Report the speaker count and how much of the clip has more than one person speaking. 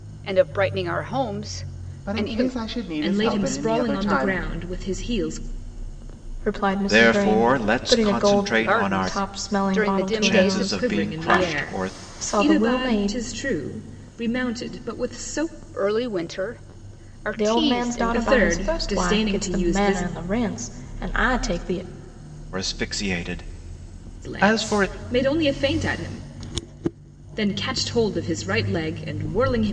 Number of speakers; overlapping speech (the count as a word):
five, about 39%